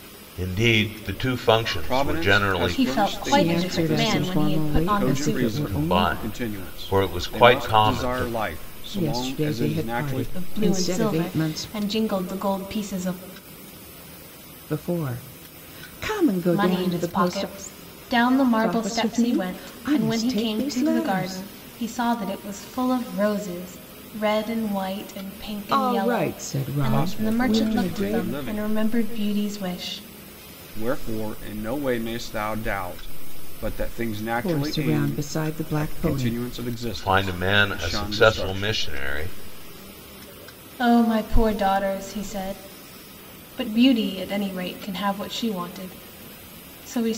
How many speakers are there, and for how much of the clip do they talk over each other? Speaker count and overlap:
four, about 43%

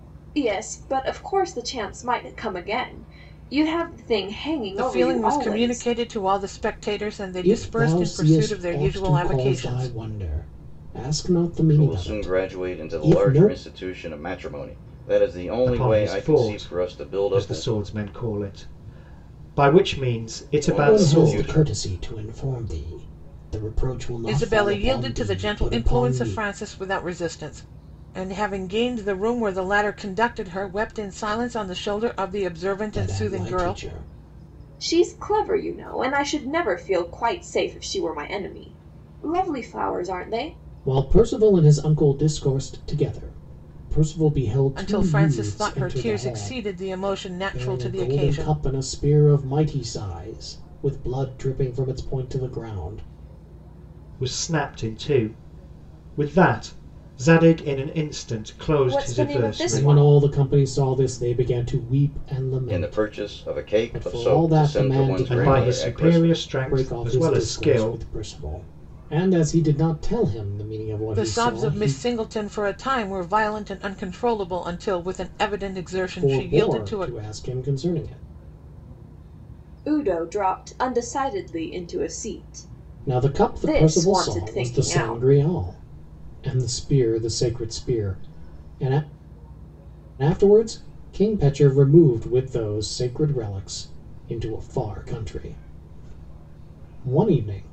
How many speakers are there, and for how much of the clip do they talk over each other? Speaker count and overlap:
five, about 26%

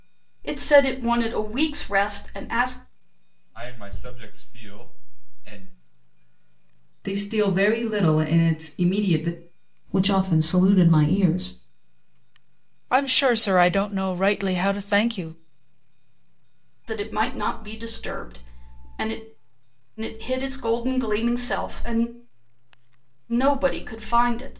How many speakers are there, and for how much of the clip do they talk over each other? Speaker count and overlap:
five, no overlap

